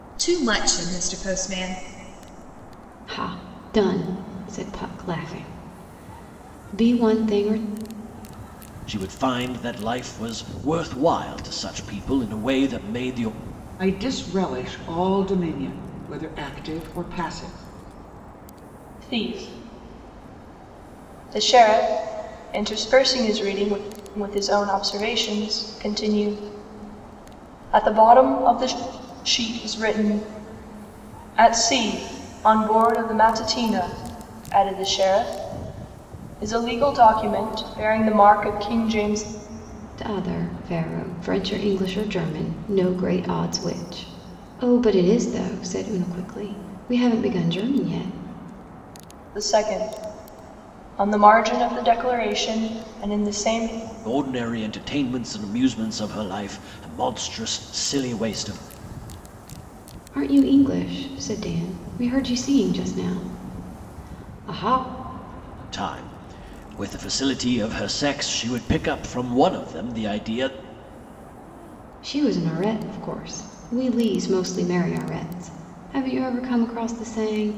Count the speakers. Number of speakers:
5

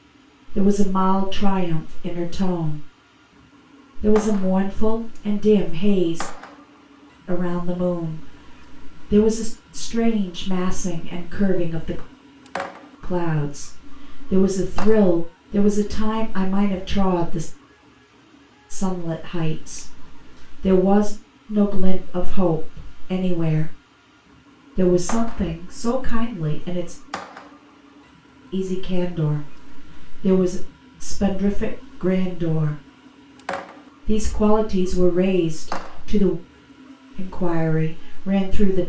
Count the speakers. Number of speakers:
1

